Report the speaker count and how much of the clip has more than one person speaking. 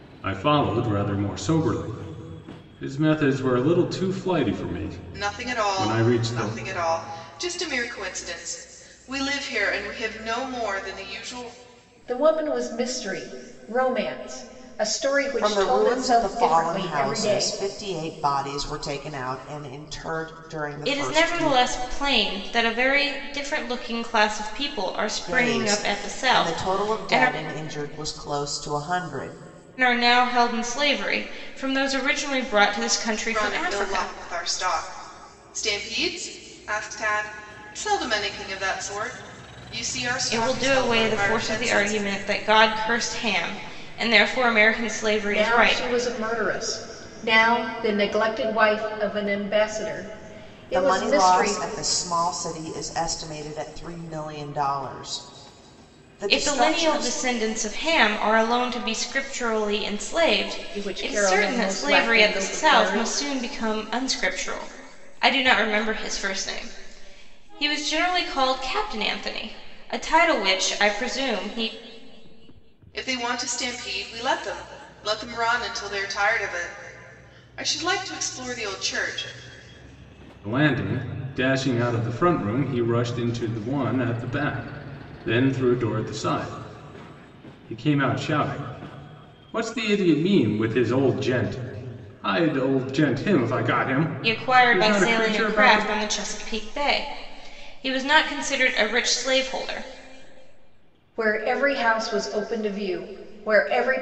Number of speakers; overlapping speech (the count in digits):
5, about 15%